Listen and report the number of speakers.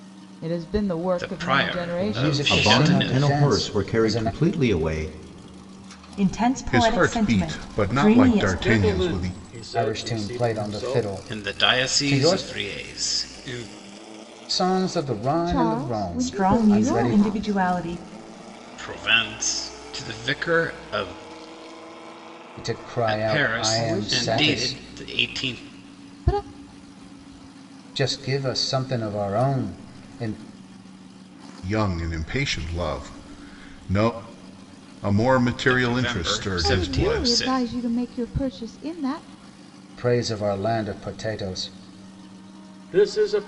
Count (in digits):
7